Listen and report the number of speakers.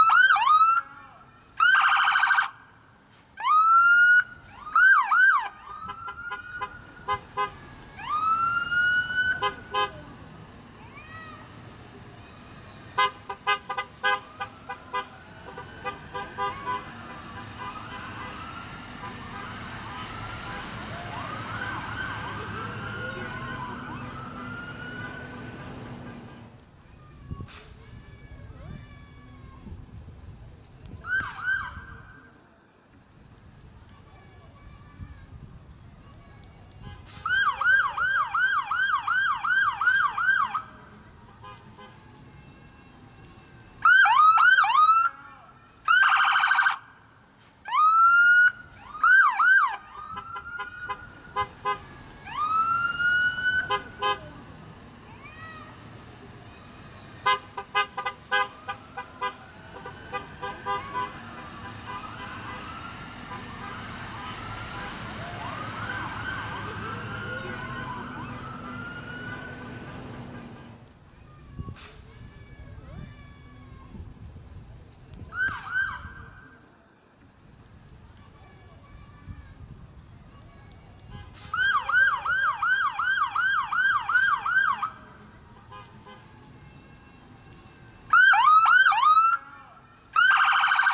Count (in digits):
0